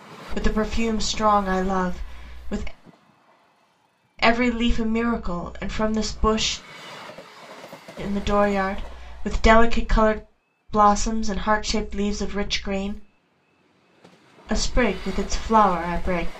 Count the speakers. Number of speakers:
1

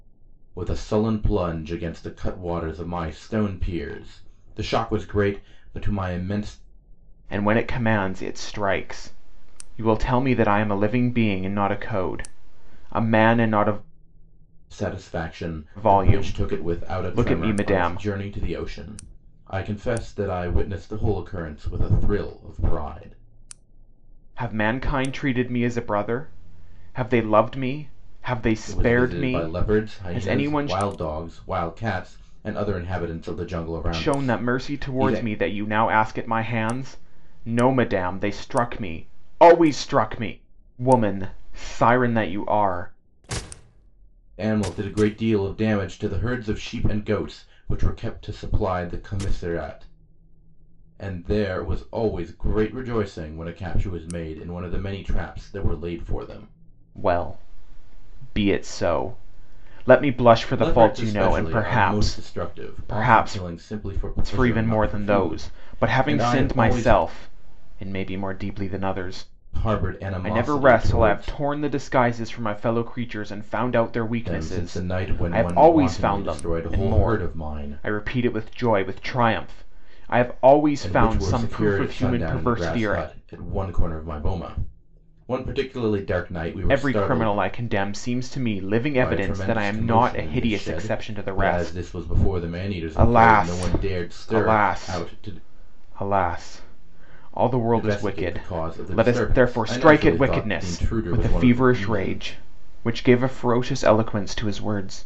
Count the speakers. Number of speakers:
2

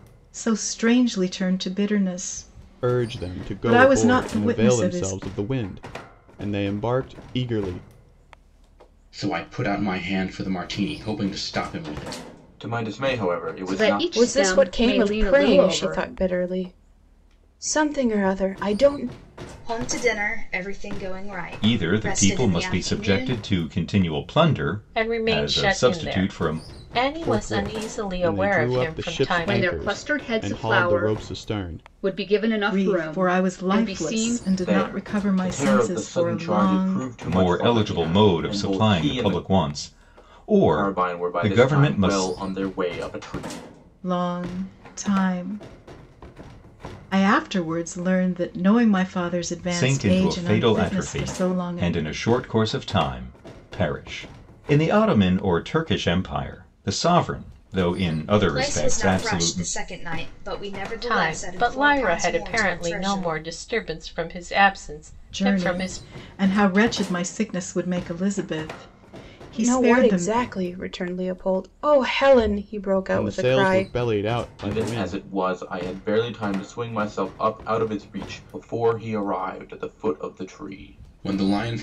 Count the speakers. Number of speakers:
8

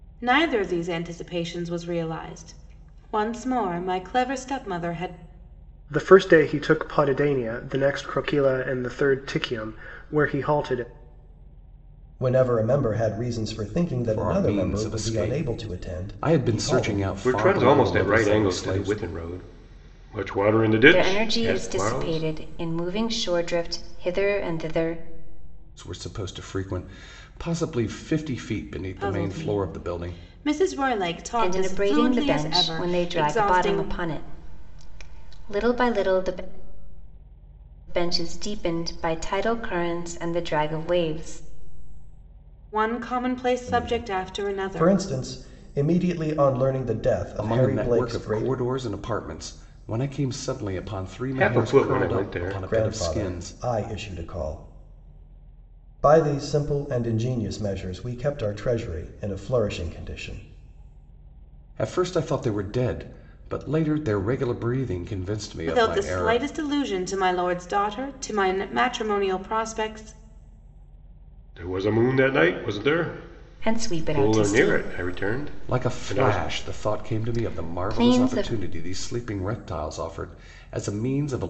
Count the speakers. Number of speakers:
6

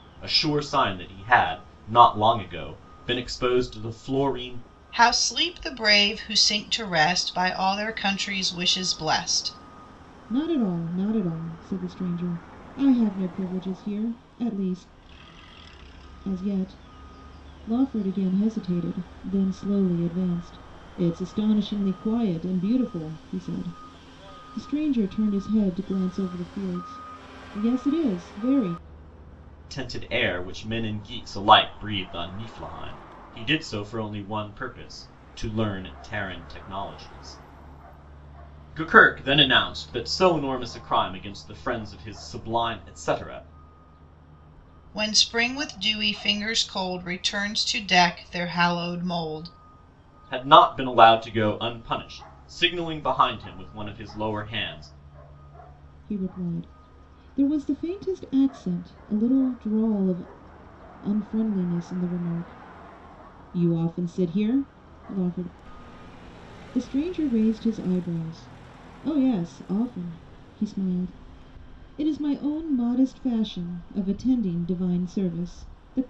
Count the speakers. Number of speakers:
3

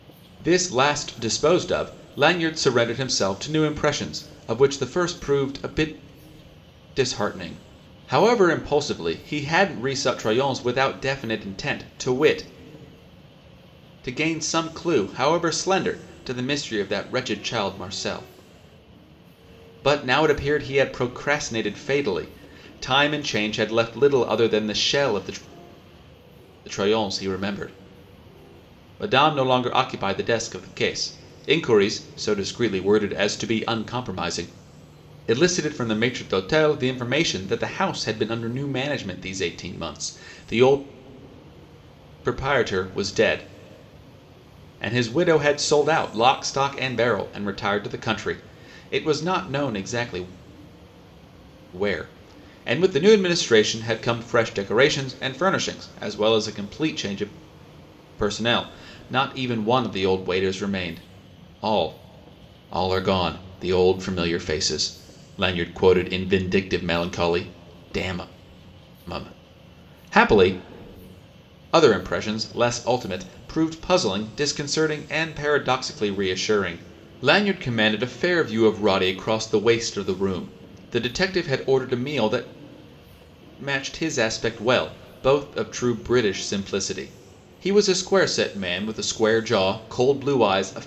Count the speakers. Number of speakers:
1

